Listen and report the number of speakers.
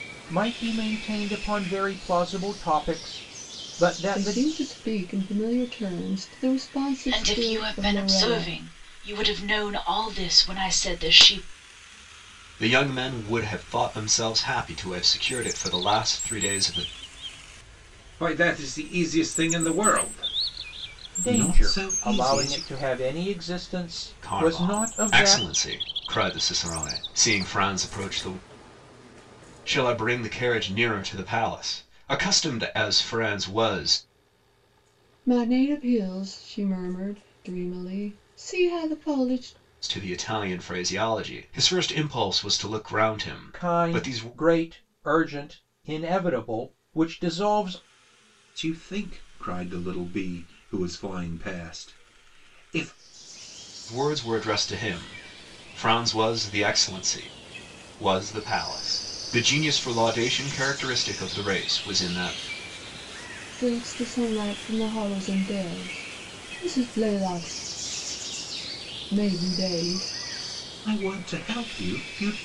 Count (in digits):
5